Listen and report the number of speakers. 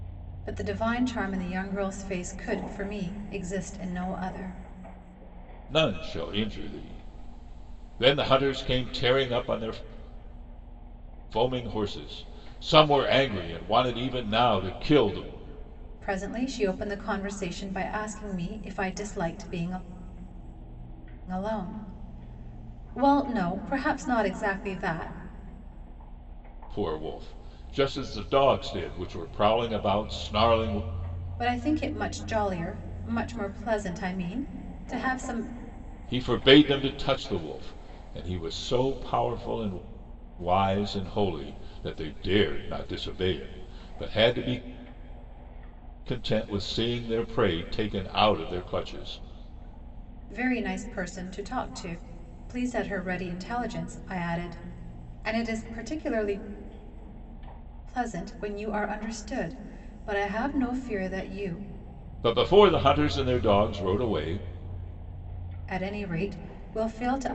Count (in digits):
2